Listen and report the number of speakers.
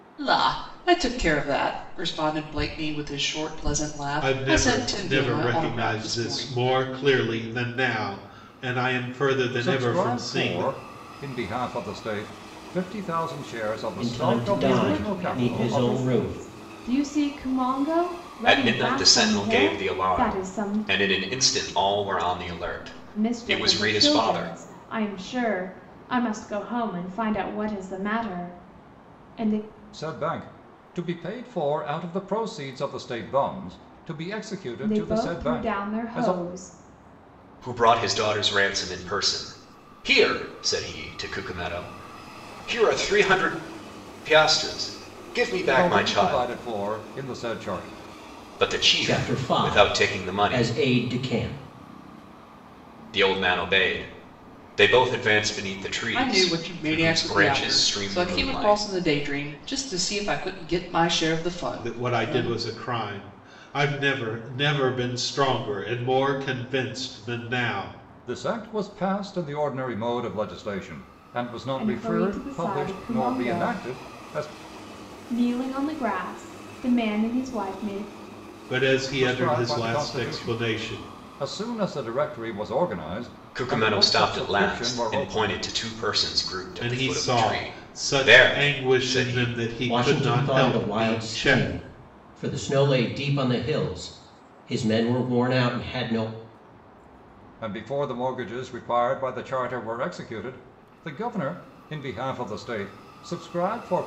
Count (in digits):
6